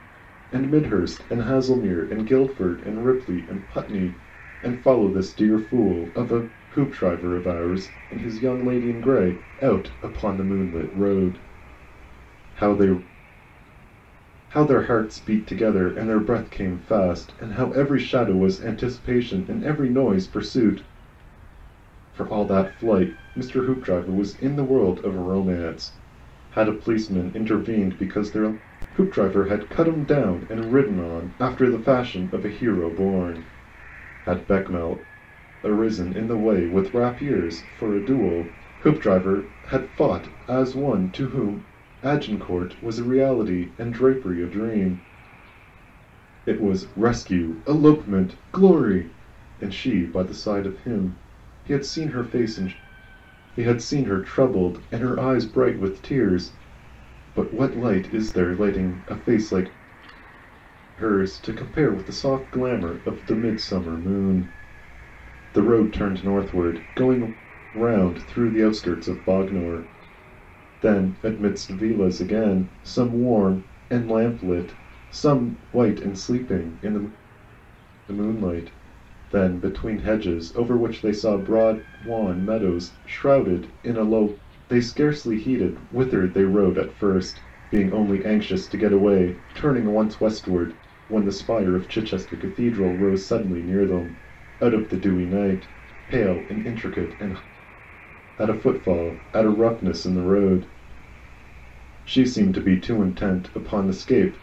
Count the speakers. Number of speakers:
one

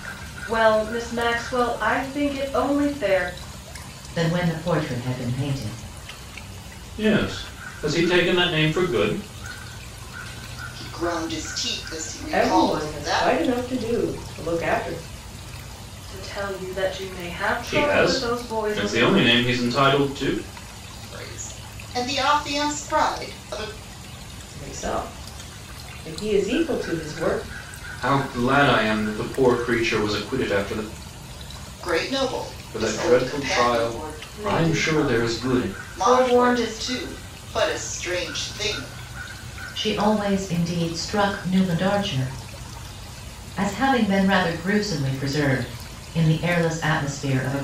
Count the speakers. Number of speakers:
five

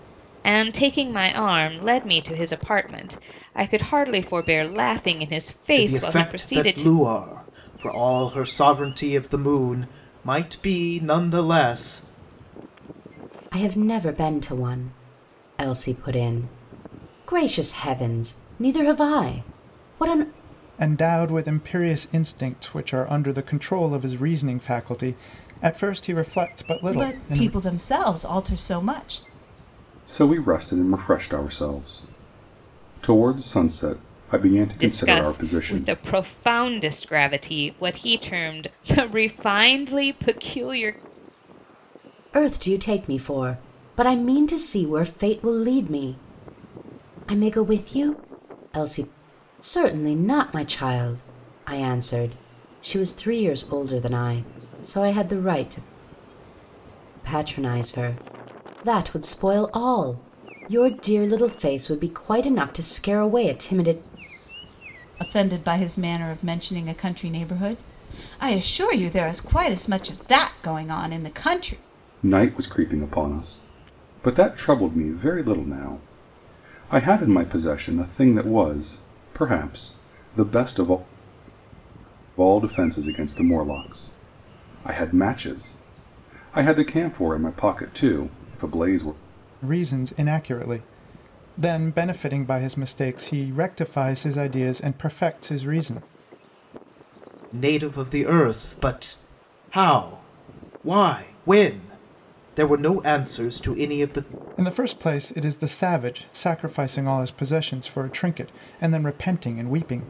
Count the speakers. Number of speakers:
six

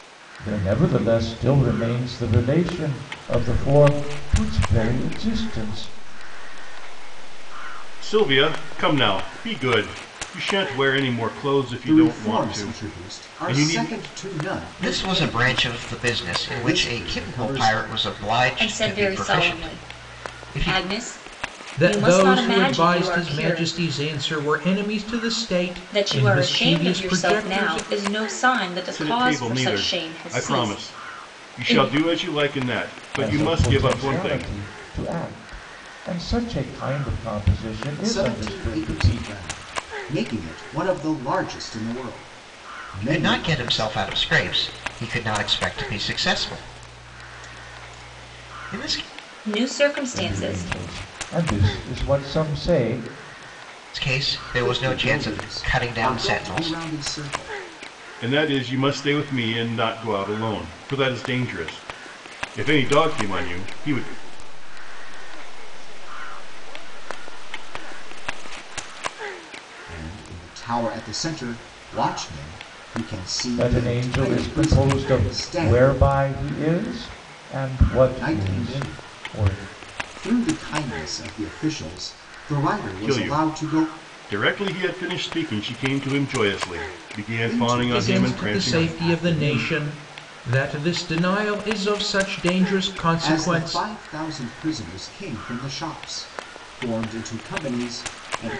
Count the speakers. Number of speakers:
seven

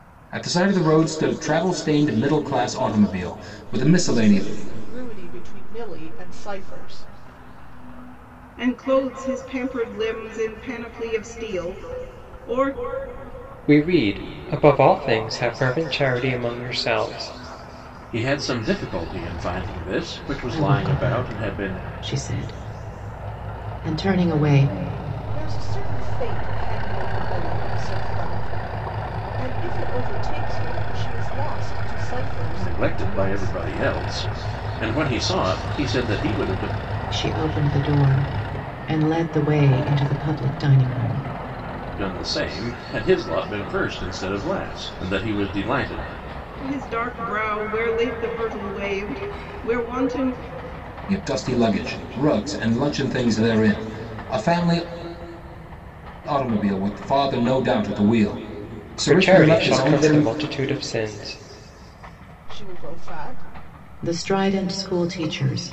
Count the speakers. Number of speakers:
six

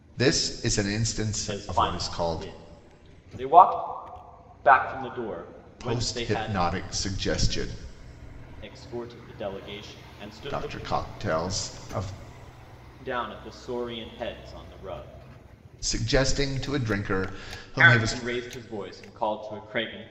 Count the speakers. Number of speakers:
two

